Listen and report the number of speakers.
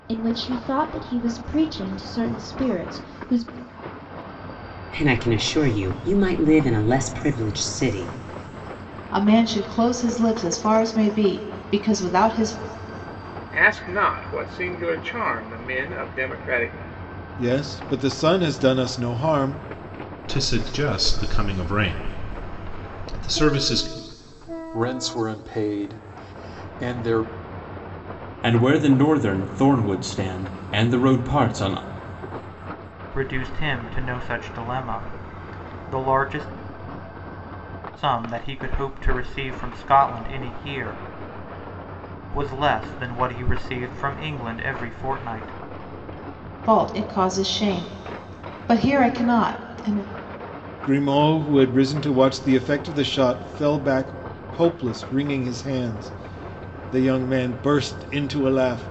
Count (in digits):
9